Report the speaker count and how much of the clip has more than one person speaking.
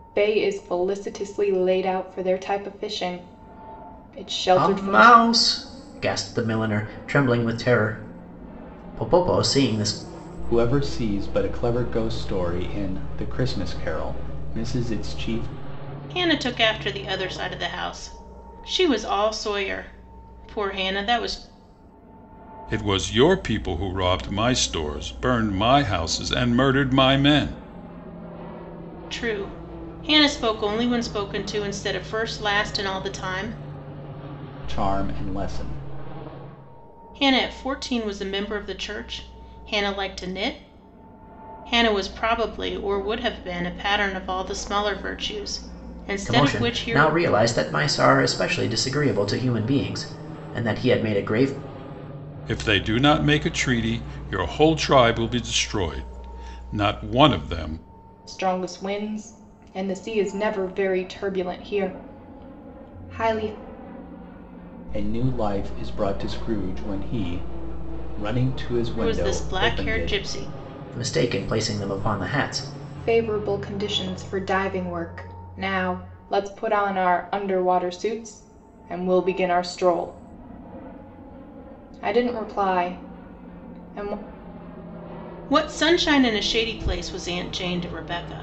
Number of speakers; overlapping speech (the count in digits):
5, about 3%